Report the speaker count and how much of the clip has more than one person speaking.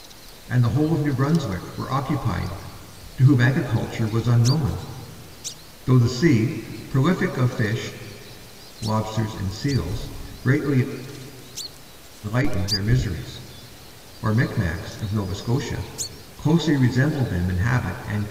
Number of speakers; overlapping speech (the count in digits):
1, no overlap